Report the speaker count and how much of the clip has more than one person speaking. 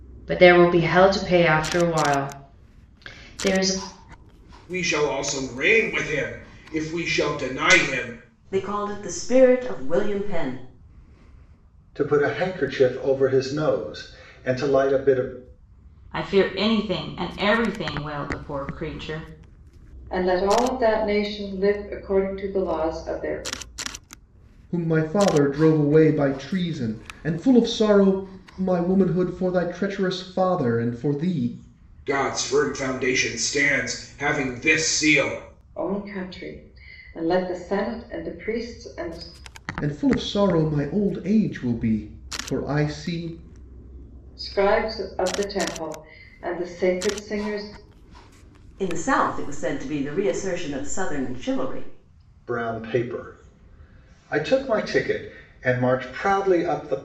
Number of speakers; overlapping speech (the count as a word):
seven, no overlap